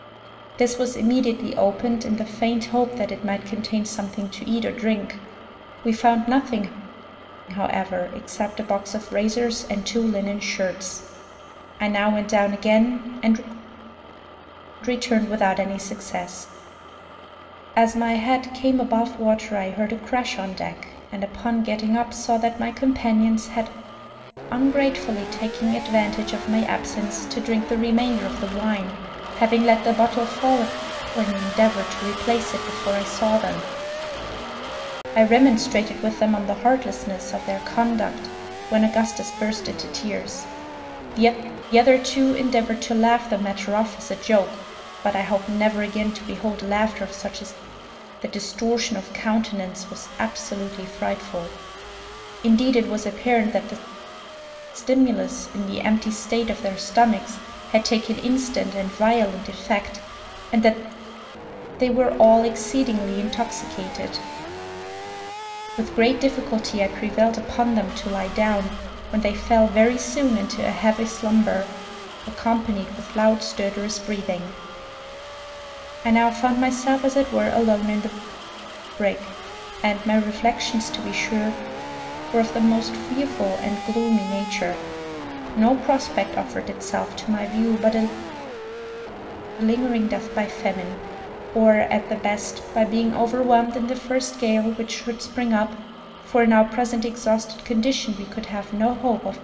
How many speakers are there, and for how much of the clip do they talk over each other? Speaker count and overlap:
one, no overlap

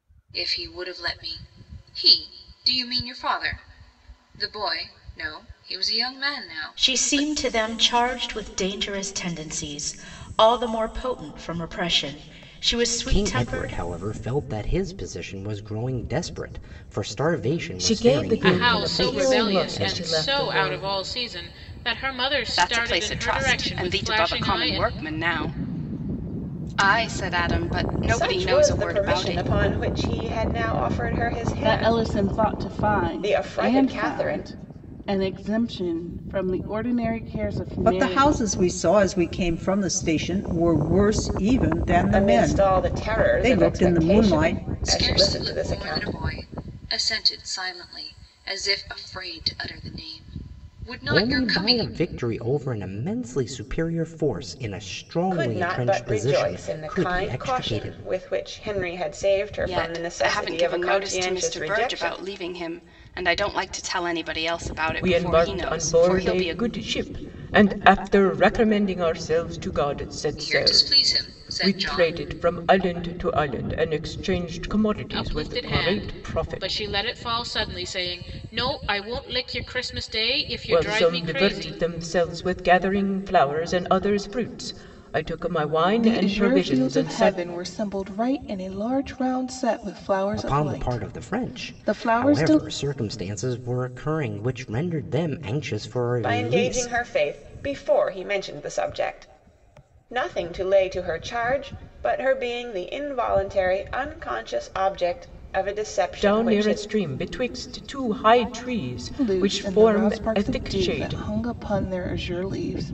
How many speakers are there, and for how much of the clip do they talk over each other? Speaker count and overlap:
nine, about 32%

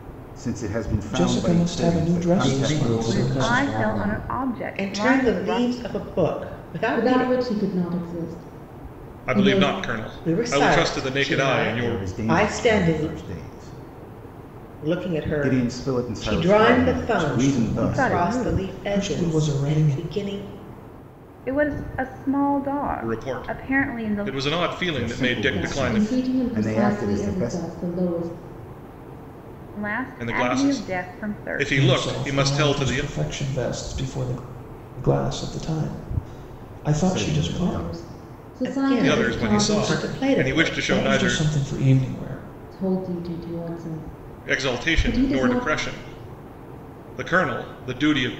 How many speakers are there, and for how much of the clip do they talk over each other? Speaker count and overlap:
seven, about 51%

